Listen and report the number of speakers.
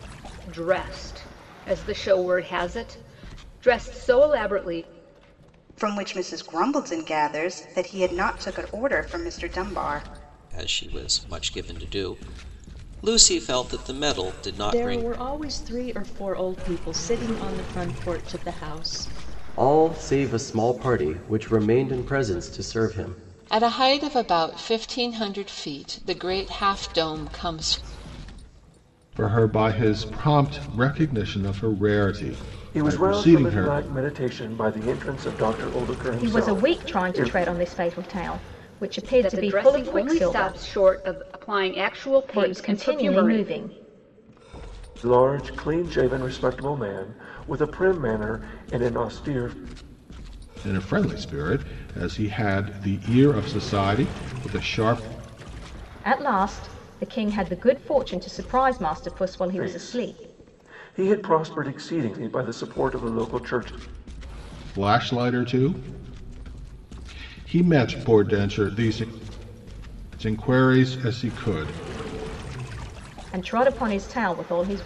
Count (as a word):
nine